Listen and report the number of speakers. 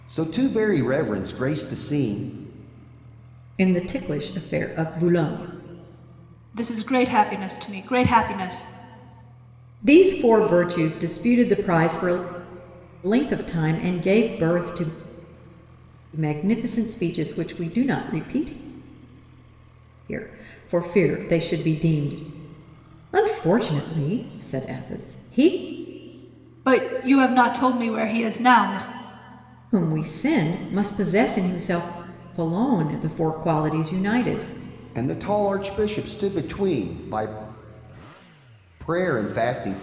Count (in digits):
3